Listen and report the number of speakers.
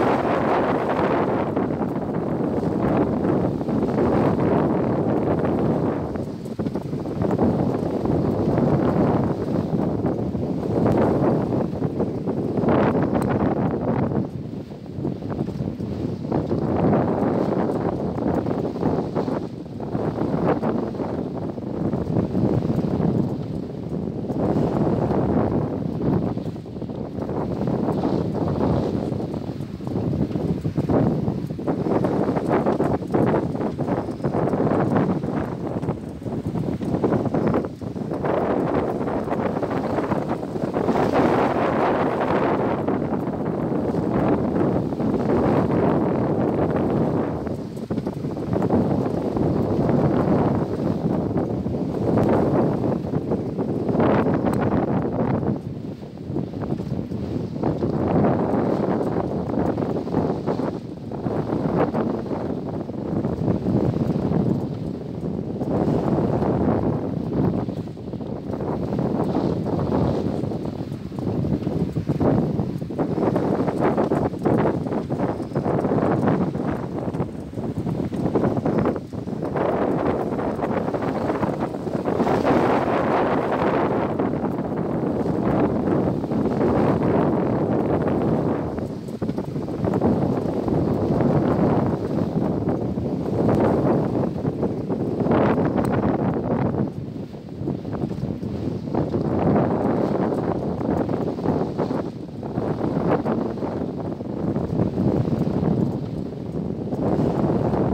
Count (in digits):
0